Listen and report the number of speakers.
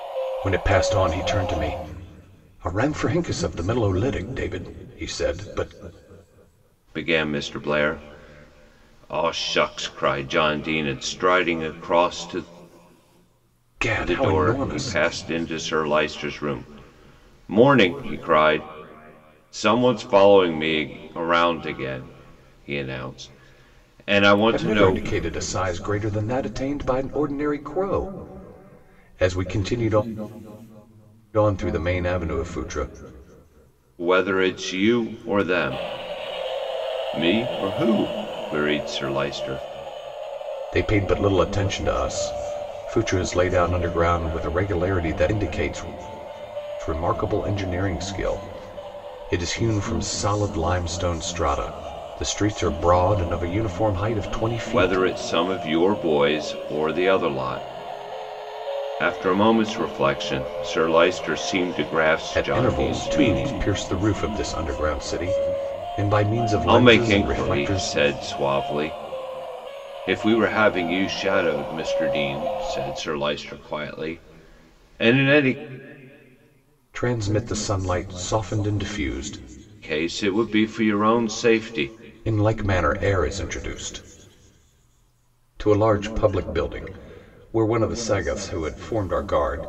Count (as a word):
two